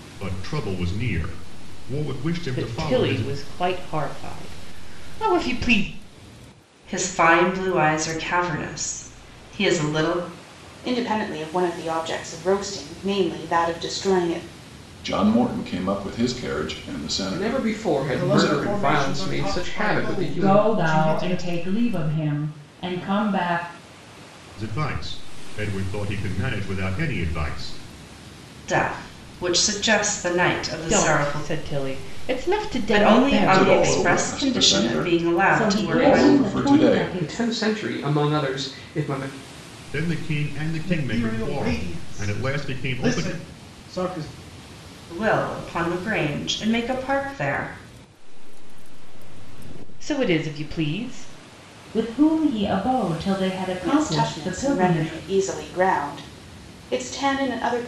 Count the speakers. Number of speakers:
9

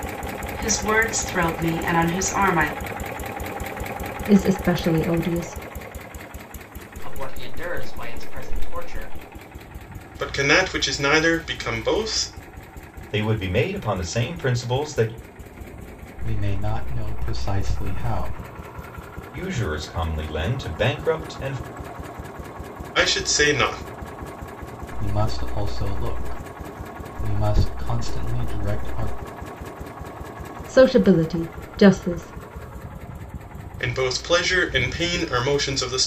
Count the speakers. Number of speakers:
6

